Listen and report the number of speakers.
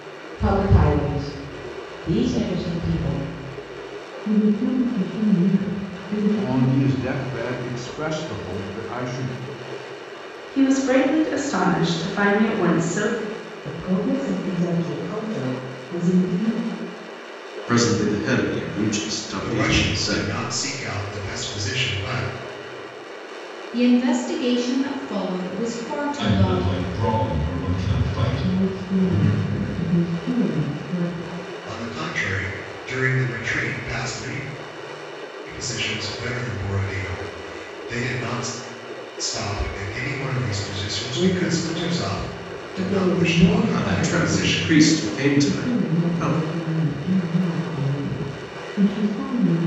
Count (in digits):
9